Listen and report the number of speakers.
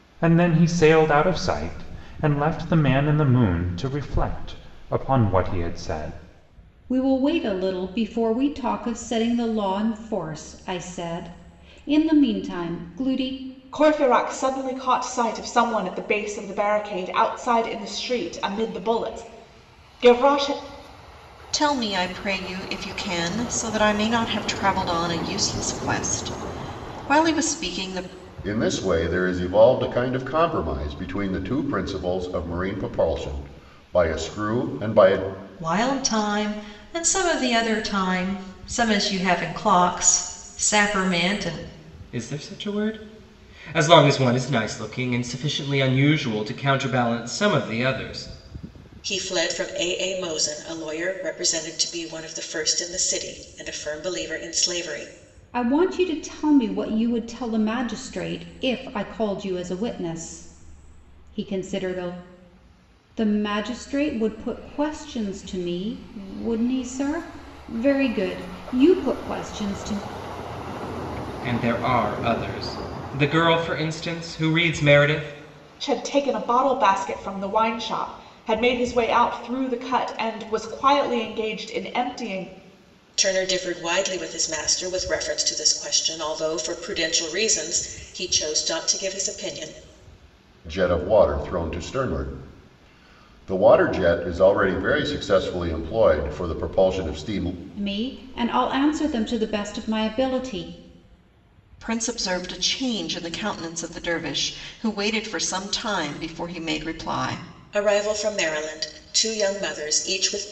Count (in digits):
8